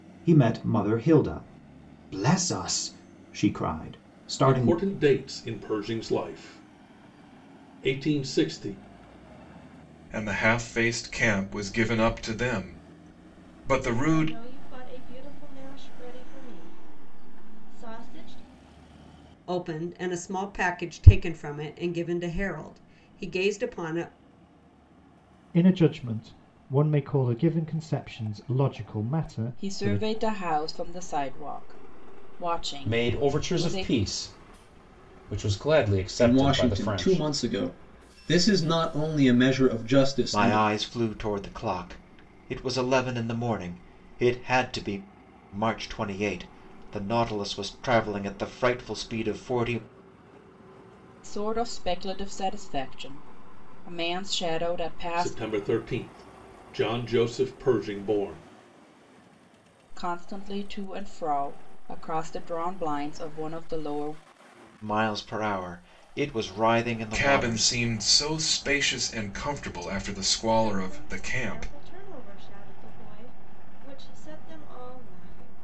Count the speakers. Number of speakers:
10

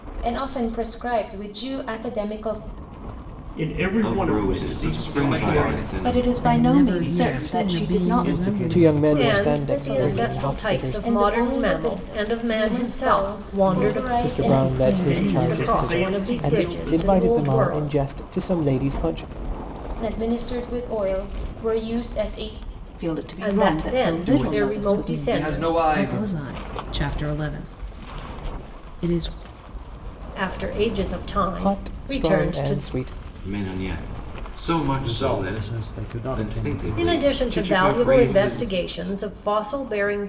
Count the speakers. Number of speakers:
9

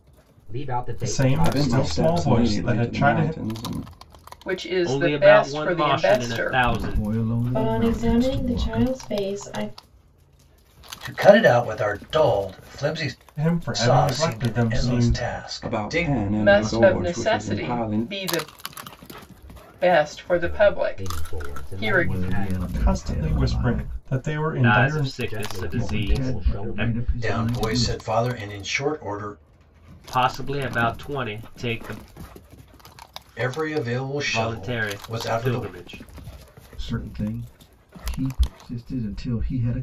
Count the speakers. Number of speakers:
8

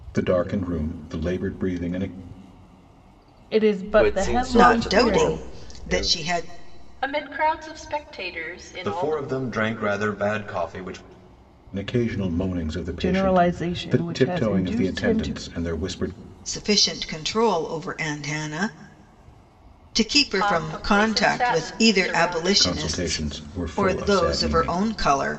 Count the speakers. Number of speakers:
6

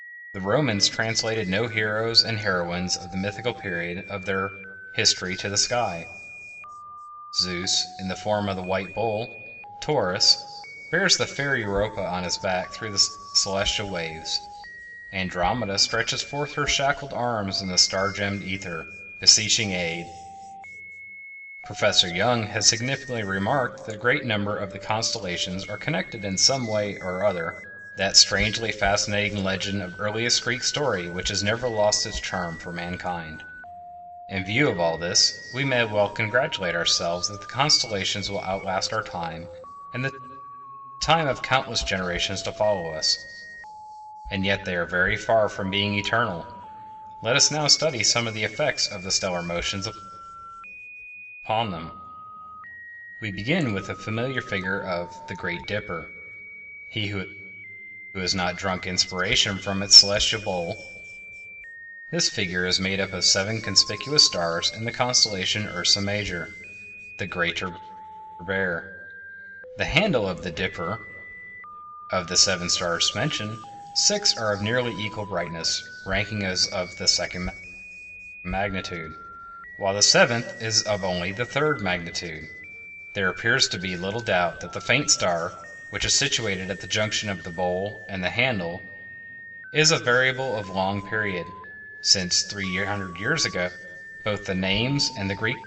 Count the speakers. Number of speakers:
1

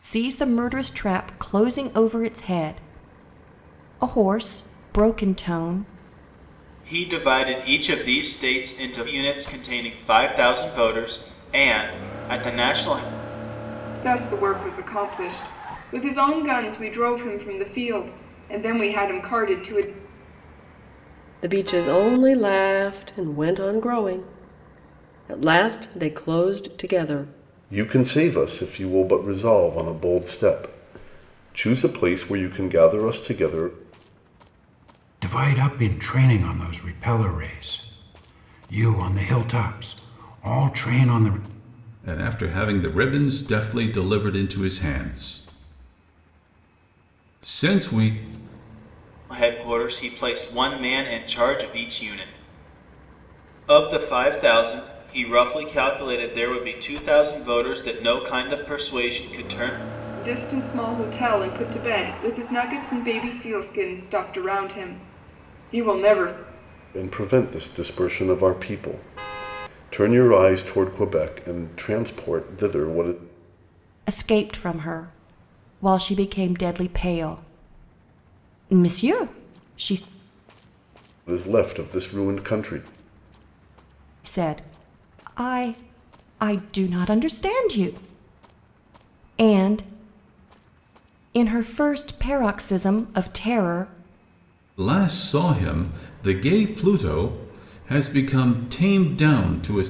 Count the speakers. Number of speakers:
7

